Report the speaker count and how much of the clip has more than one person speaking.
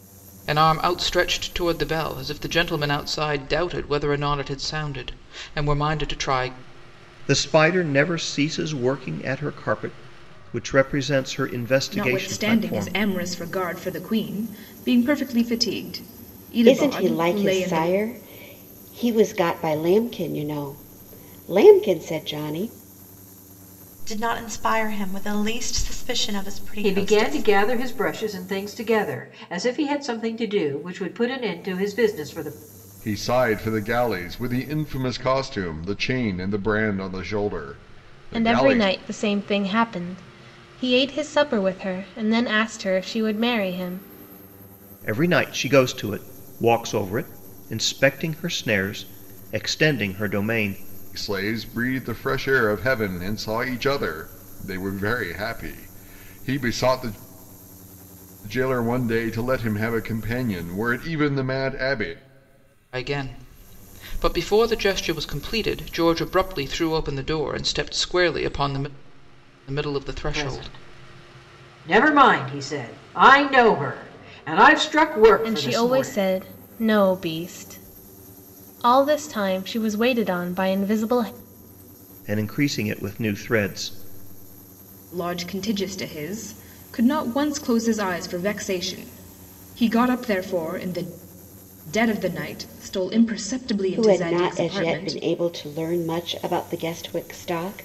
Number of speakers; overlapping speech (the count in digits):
8, about 7%